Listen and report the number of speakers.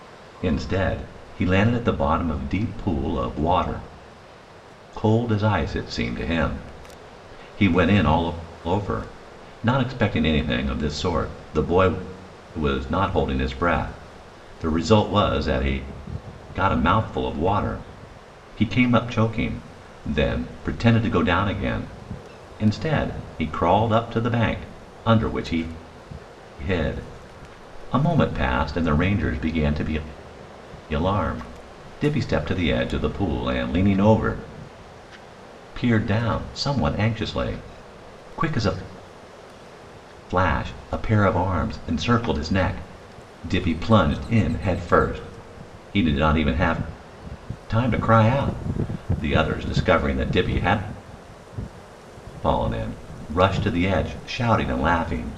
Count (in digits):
1